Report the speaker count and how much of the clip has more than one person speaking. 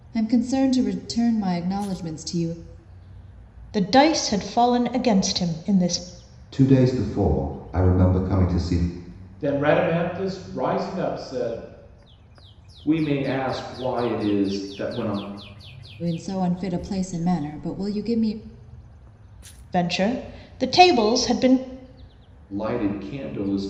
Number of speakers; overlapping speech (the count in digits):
5, no overlap